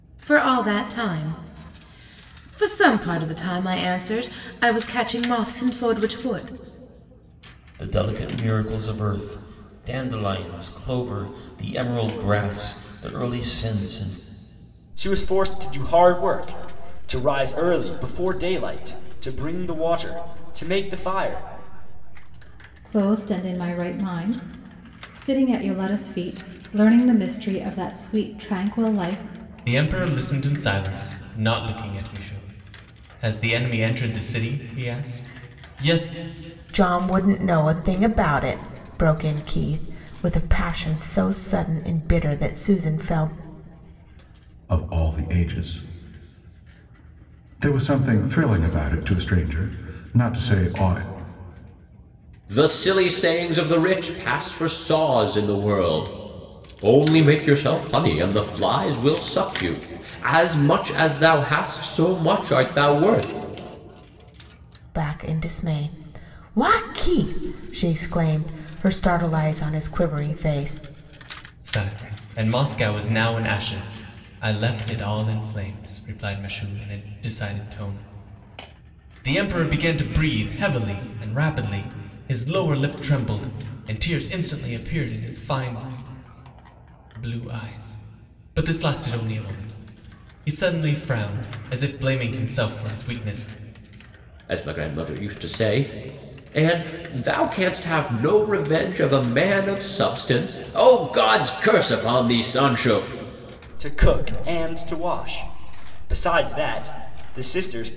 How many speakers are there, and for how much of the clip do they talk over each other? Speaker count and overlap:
8, no overlap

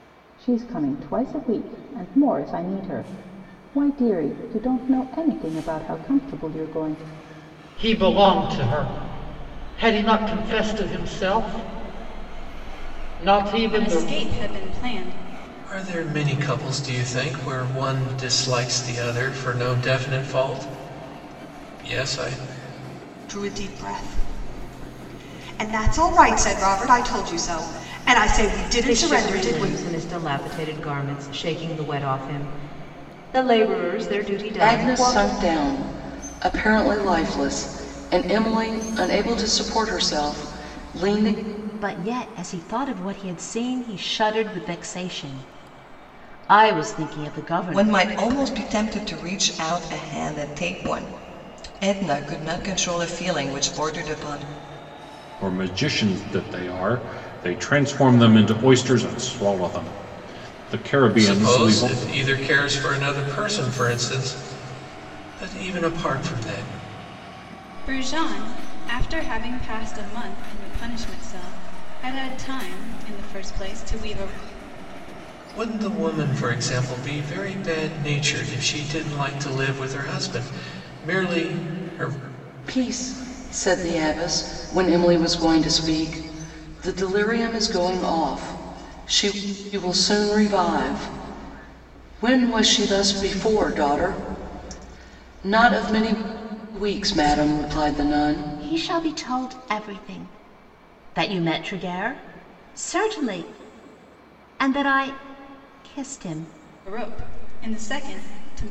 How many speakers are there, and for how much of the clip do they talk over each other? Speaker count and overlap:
10, about 4%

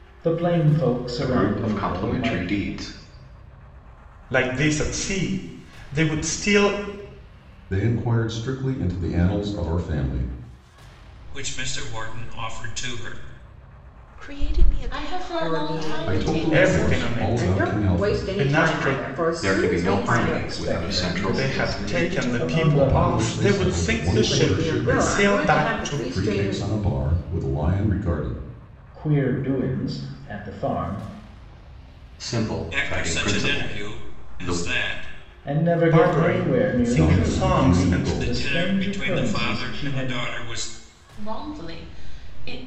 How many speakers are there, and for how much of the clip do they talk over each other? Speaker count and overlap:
8, about 45%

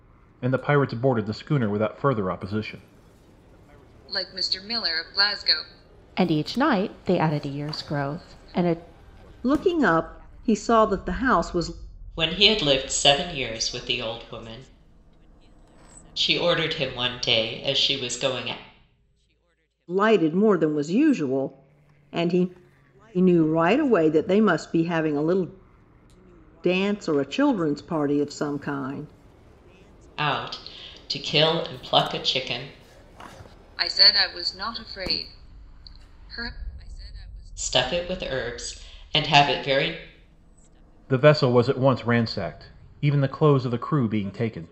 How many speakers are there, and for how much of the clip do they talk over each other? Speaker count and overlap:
5, no overlap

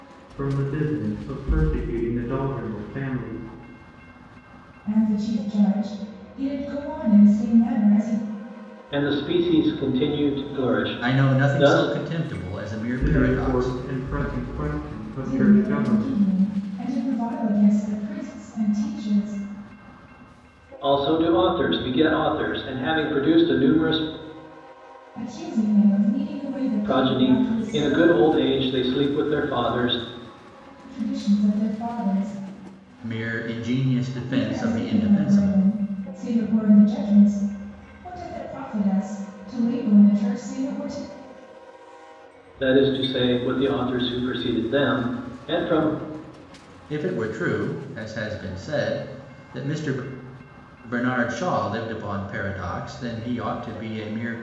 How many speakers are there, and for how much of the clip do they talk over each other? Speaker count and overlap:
4, about 11%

